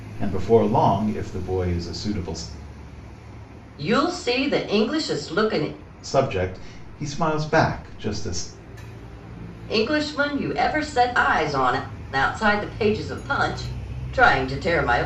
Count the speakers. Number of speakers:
2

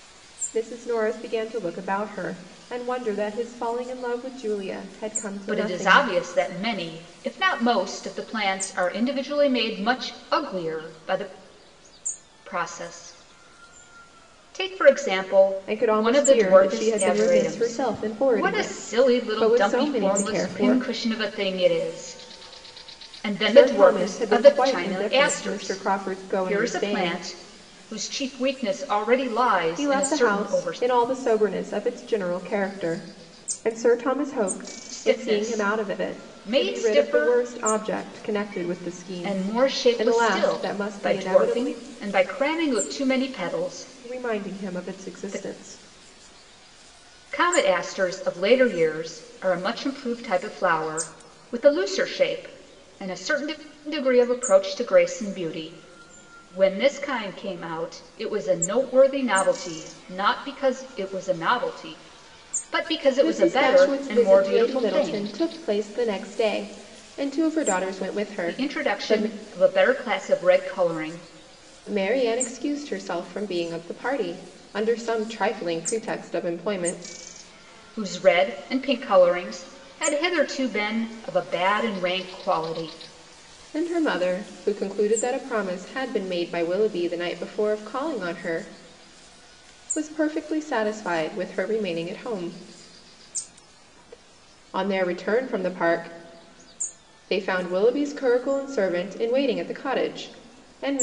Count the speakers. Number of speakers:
2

